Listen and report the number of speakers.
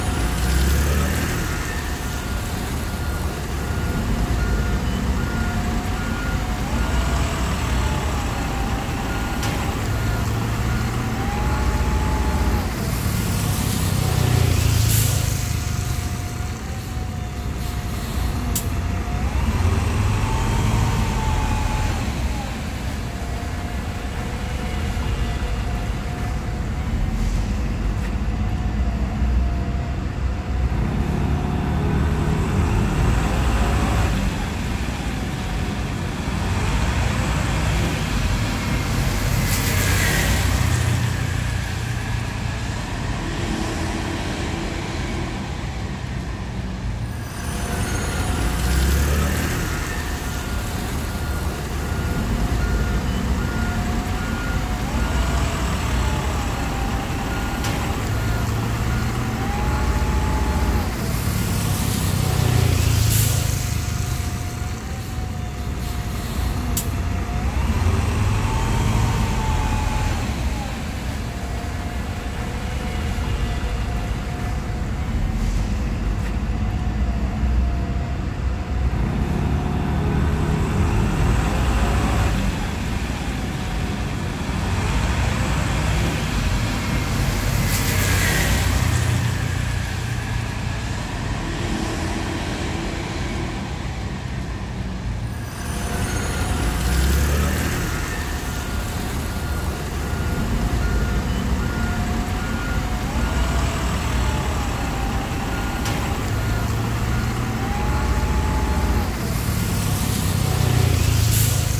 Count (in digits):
0